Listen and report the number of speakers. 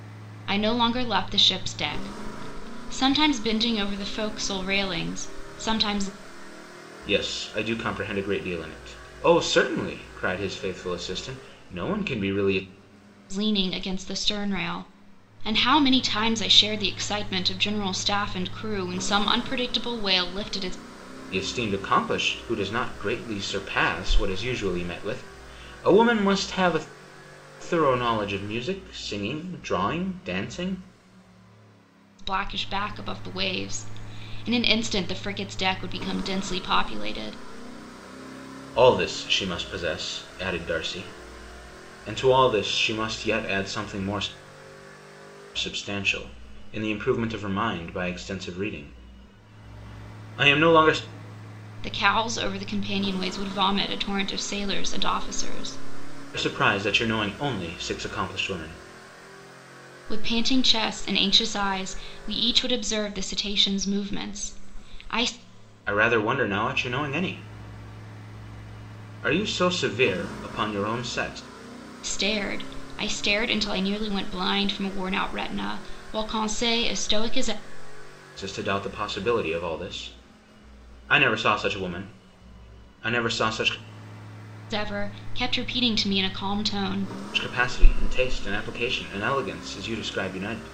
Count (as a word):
two